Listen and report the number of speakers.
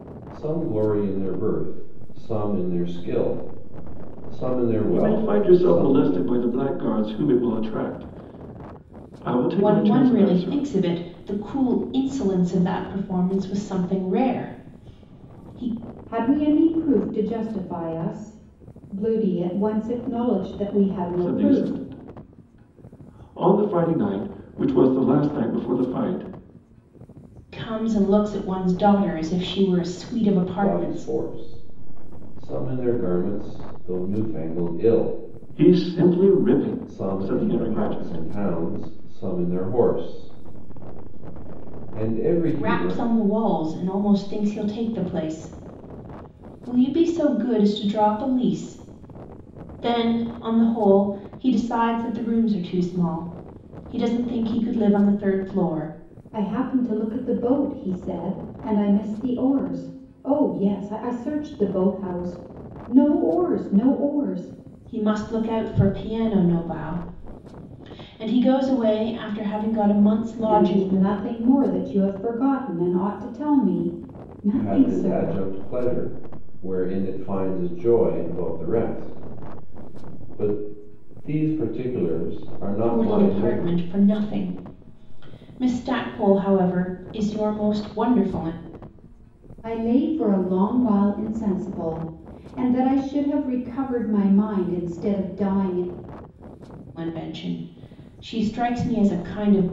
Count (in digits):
4